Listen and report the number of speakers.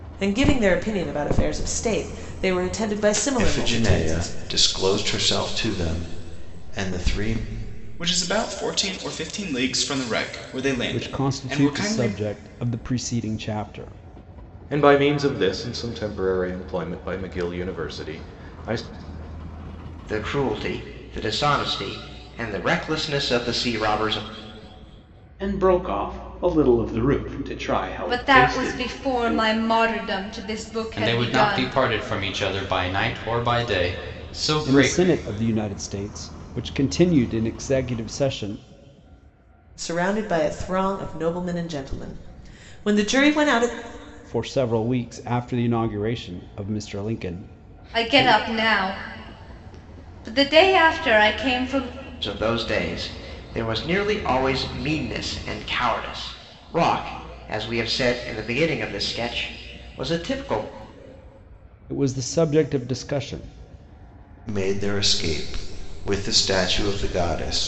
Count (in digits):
9